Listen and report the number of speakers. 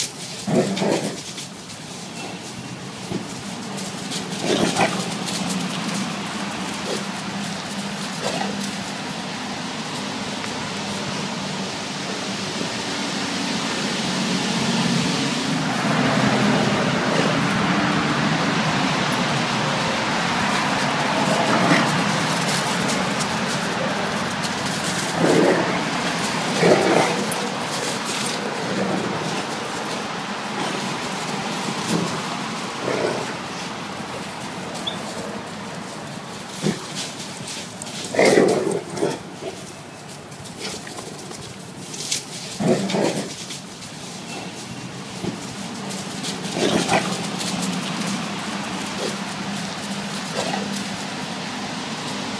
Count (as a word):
zero